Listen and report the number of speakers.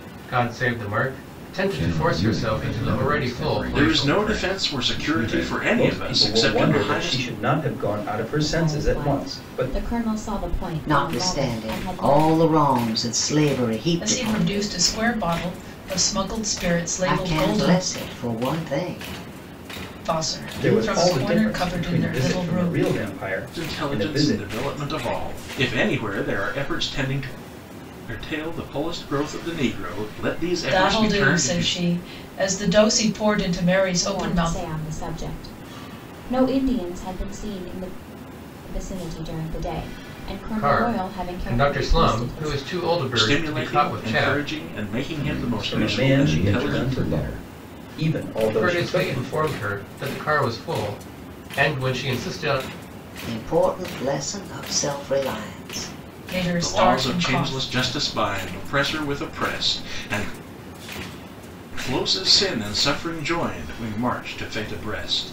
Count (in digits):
7